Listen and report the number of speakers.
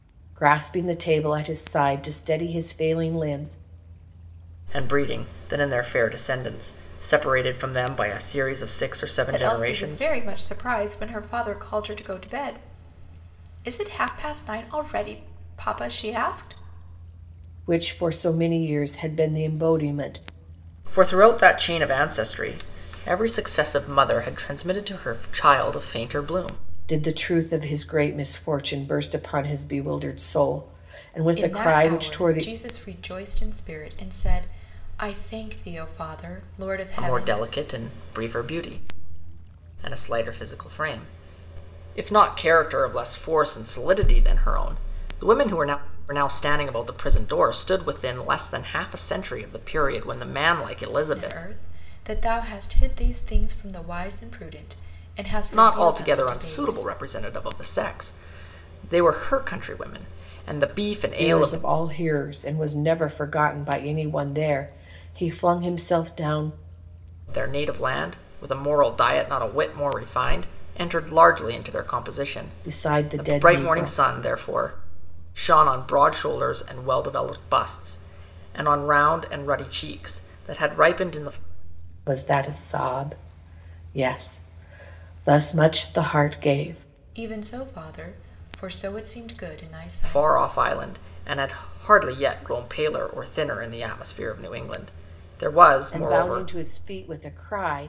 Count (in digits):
3